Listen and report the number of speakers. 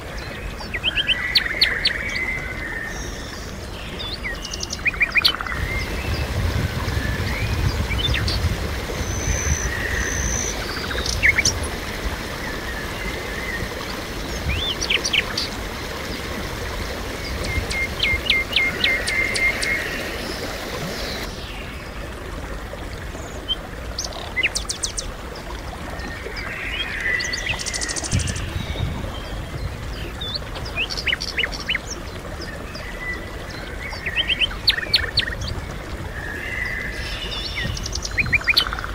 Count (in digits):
0